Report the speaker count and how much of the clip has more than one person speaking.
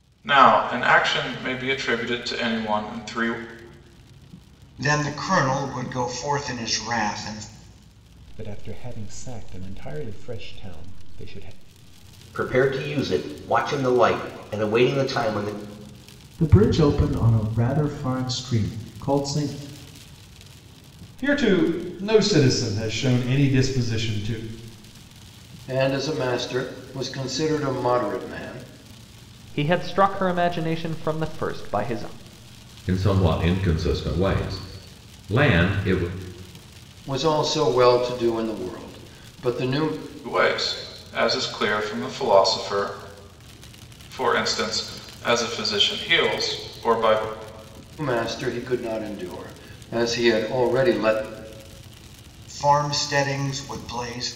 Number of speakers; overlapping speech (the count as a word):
nine, no overlap